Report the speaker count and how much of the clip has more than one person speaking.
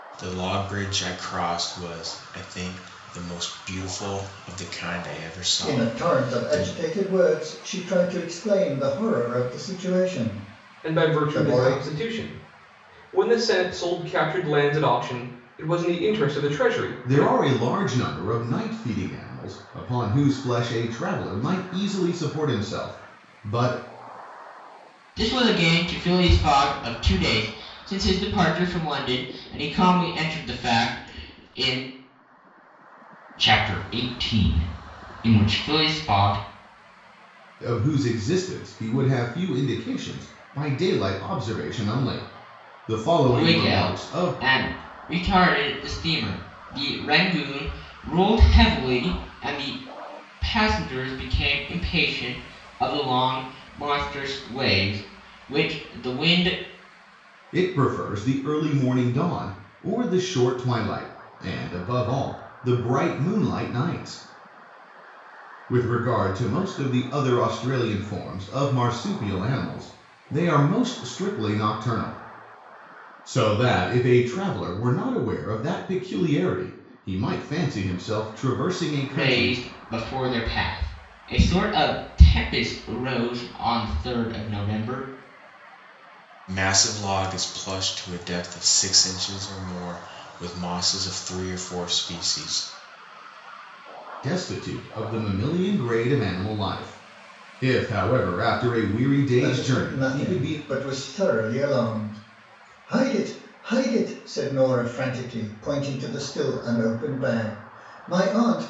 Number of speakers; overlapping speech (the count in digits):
5, about 5%